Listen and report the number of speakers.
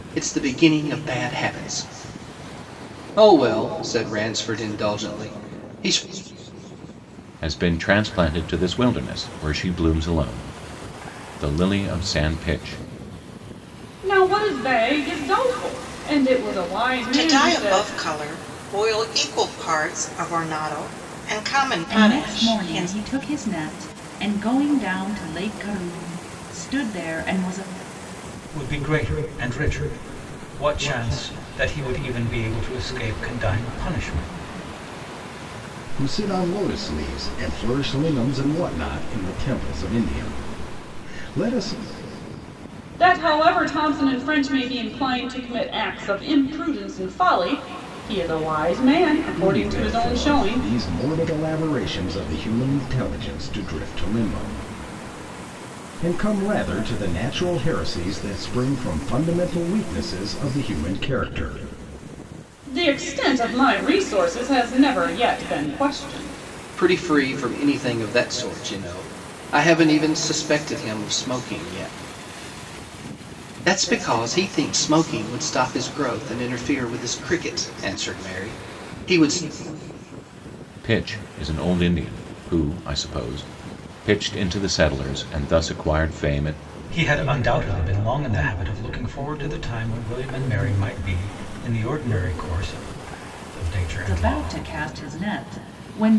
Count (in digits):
7